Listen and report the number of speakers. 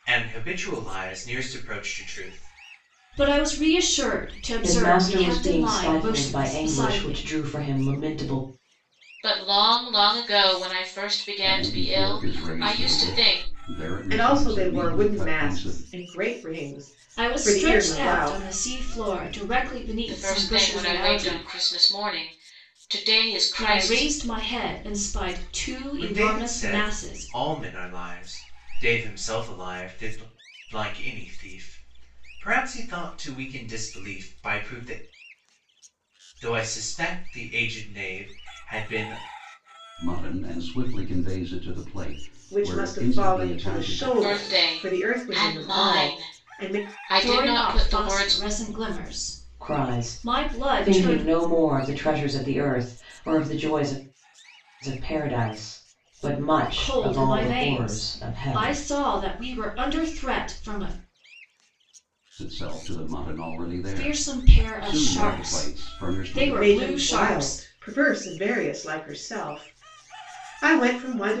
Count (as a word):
six